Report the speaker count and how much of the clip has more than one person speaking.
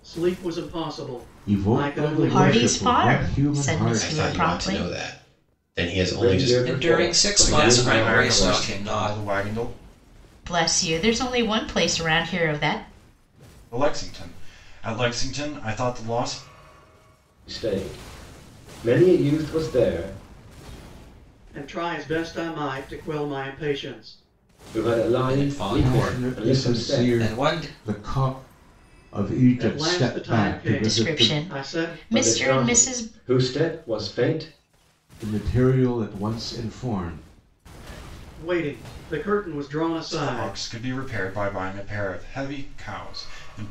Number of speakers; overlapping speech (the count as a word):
seven, about 30%